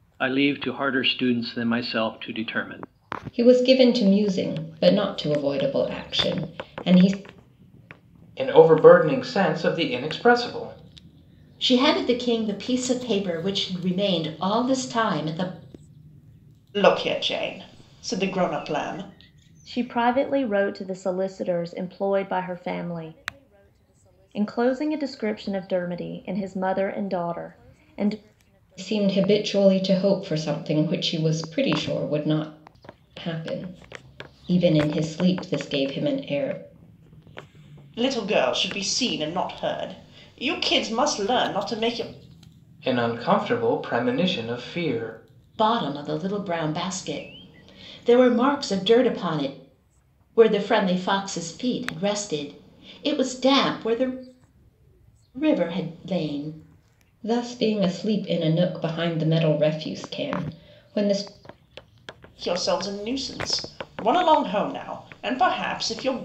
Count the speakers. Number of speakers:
6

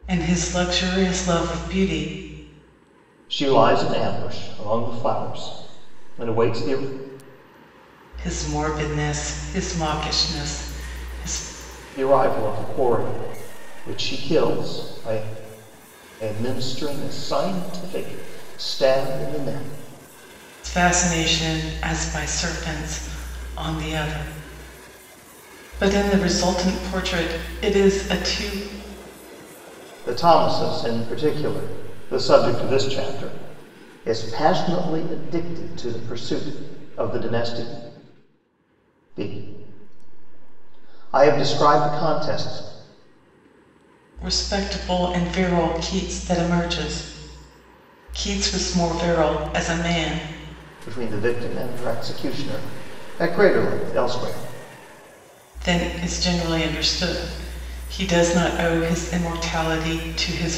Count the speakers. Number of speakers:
2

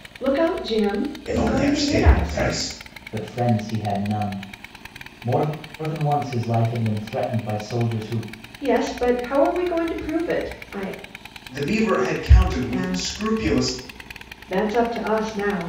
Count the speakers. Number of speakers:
3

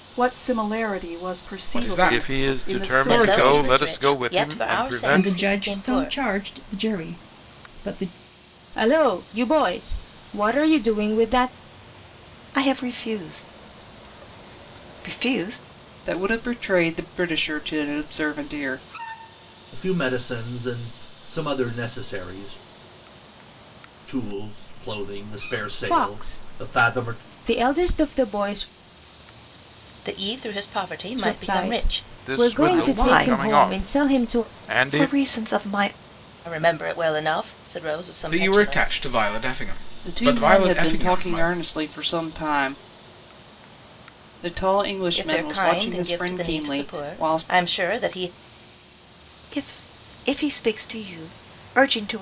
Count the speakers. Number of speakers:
9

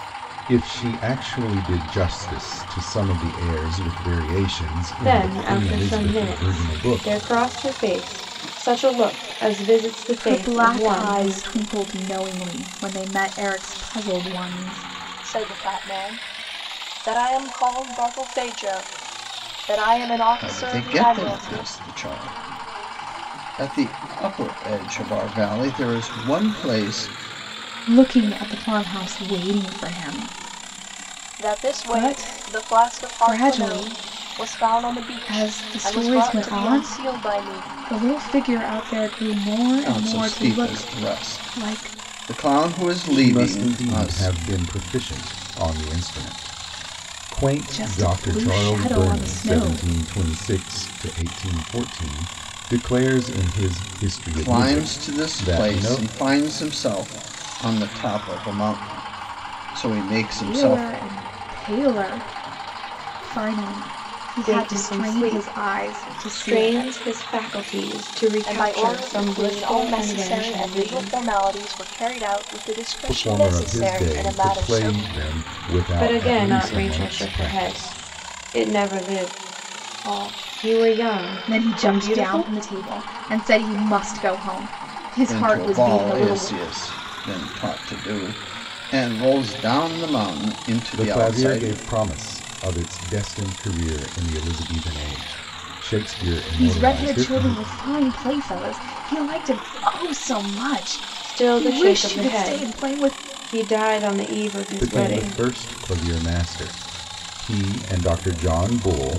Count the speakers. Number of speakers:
5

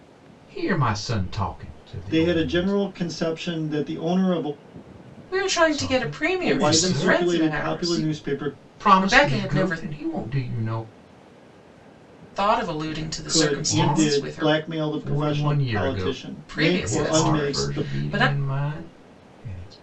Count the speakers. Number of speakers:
3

